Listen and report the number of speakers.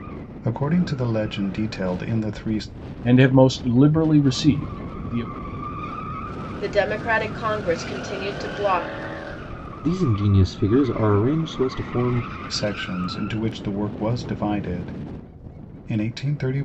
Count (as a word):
four